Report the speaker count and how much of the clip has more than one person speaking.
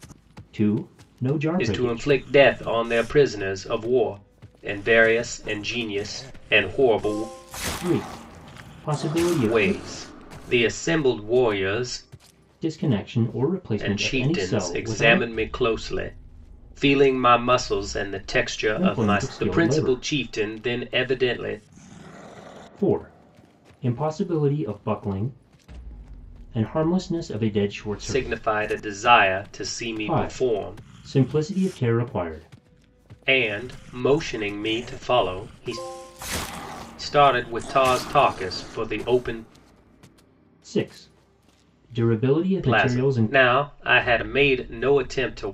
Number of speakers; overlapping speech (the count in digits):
2, about 13%